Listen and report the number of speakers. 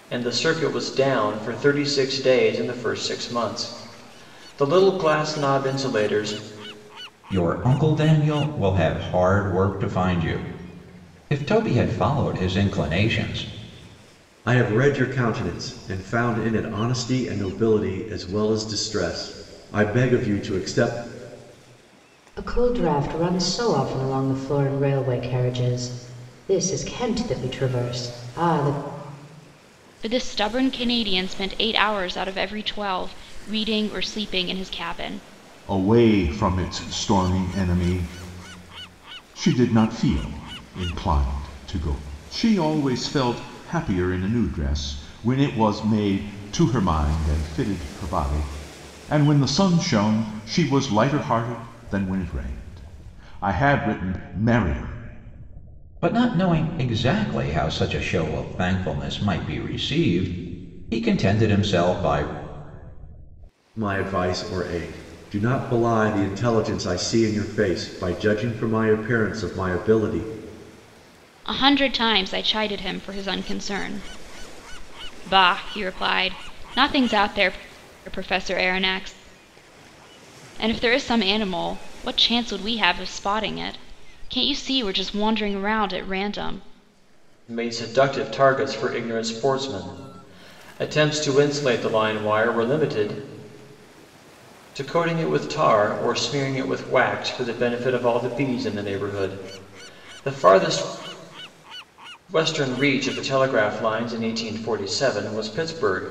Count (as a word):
six